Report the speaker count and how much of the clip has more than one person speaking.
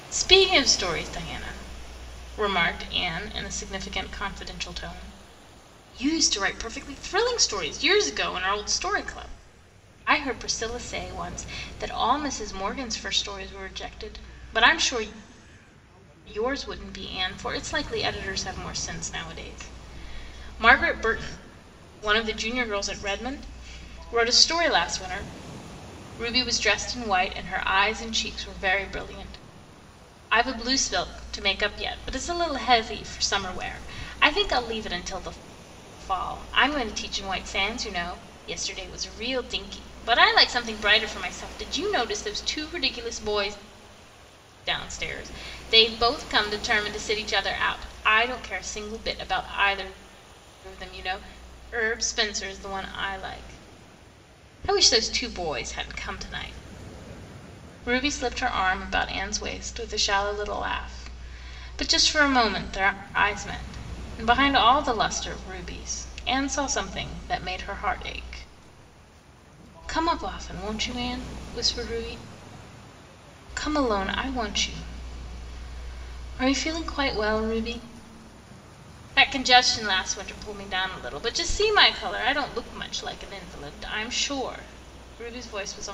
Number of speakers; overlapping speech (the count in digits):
1, no overlap